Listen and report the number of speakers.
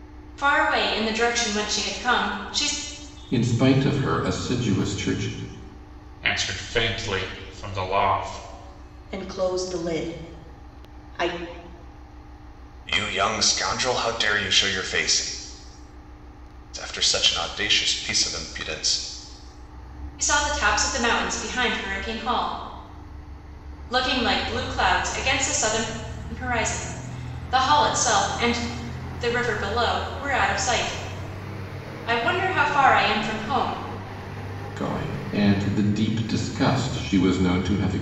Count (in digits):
5